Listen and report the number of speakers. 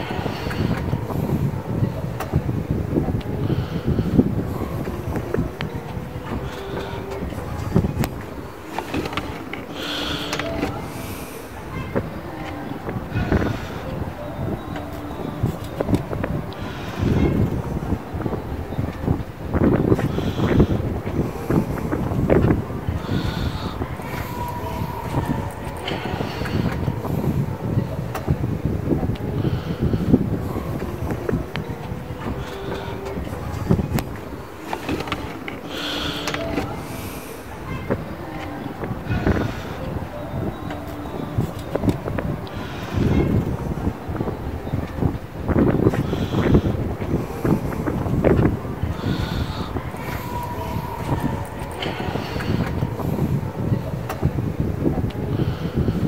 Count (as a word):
zero